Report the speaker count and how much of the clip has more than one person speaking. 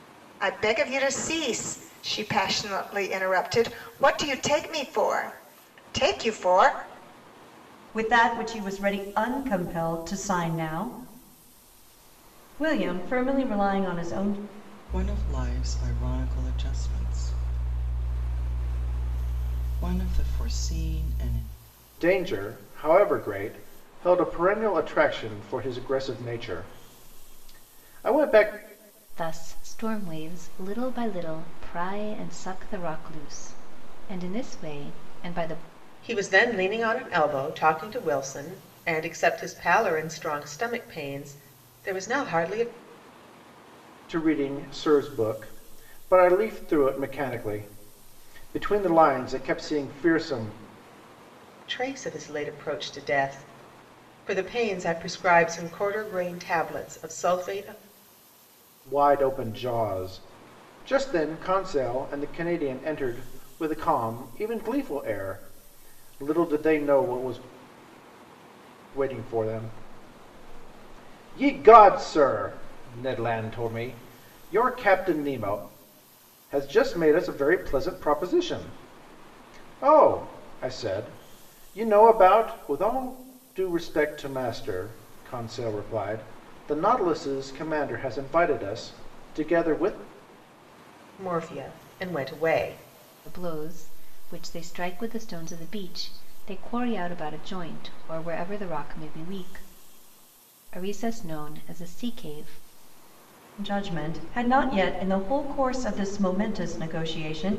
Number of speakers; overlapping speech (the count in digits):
6, no overlap